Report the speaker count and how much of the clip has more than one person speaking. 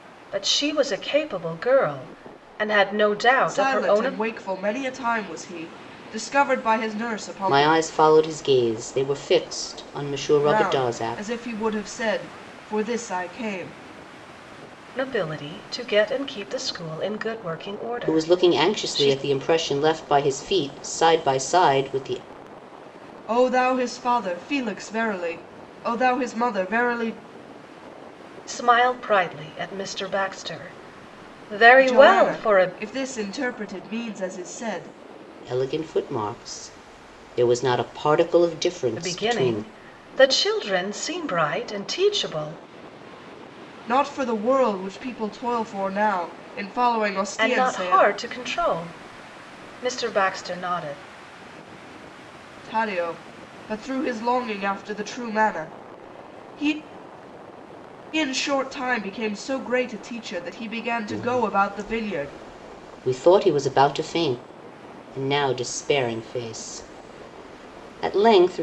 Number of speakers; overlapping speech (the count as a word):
three, about 10%